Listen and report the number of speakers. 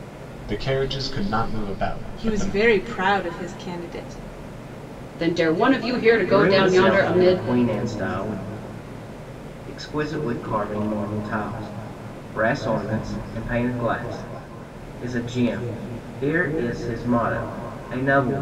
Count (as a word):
four